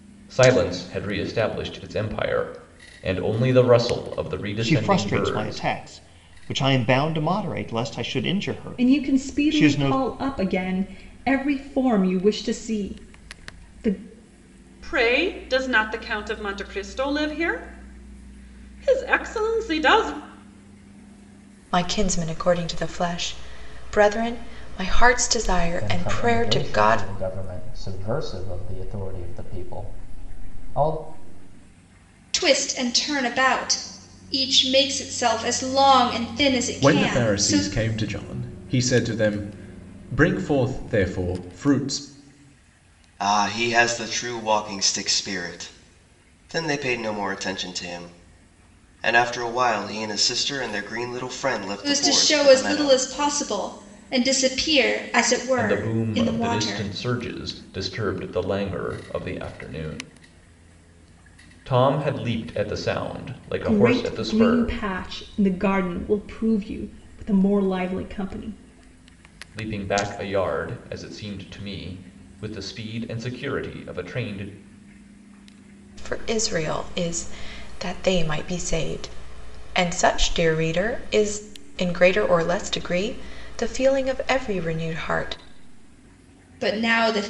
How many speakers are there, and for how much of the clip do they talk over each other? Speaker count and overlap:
9, about 9%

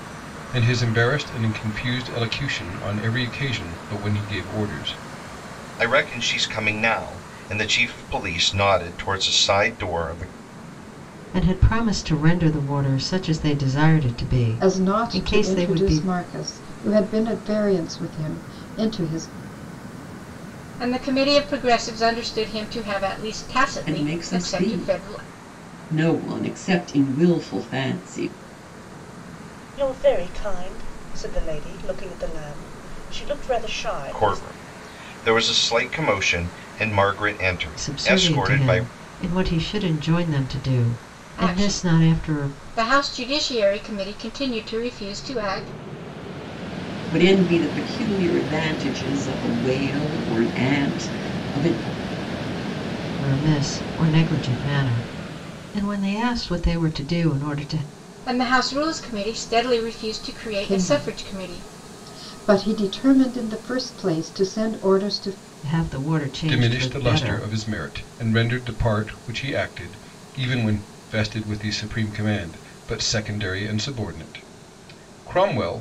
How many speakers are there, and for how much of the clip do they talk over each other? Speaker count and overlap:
7, about 10%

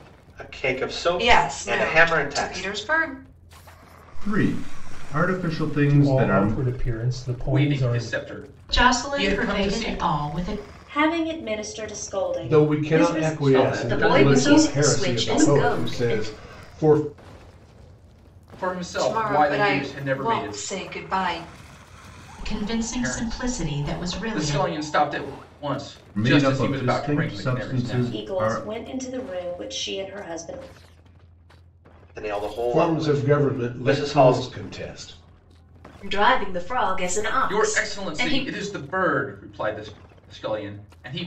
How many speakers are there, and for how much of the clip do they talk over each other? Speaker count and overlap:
10, about 42%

